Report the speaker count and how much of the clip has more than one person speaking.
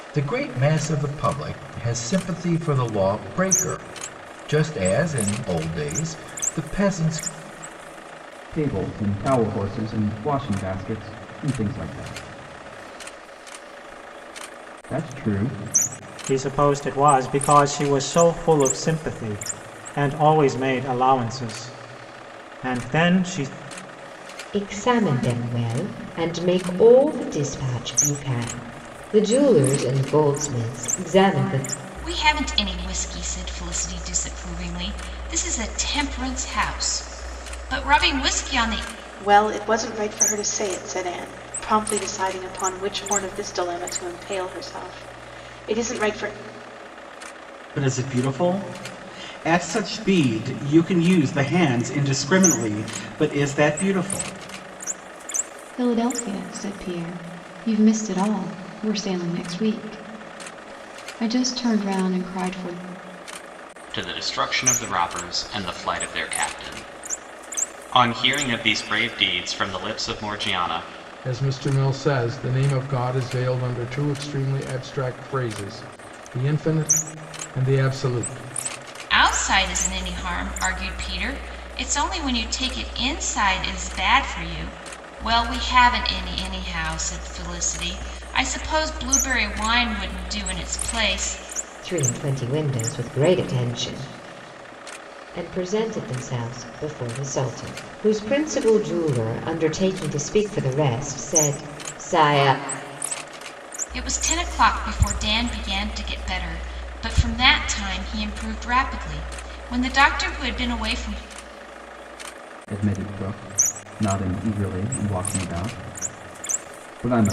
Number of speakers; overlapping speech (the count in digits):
10, no overlap